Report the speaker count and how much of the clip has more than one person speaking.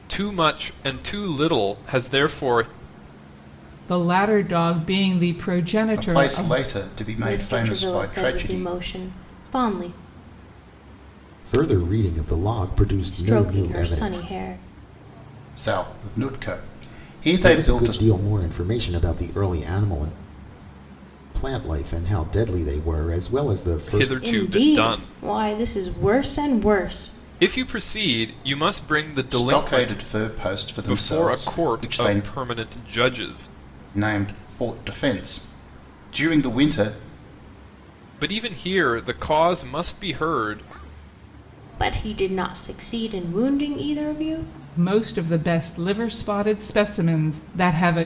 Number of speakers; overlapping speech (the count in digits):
5, about 15%